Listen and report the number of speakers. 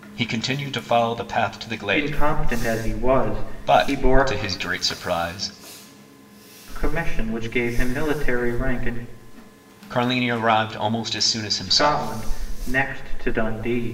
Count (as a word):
two